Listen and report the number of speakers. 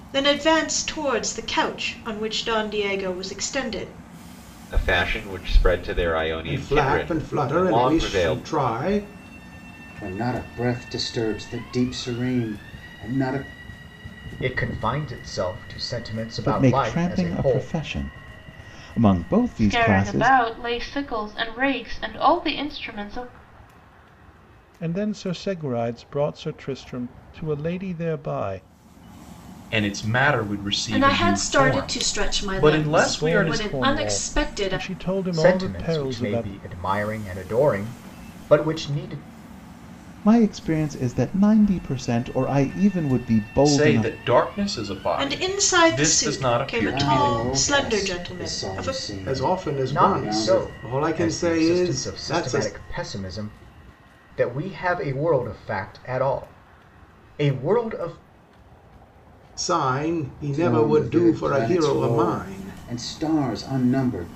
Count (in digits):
10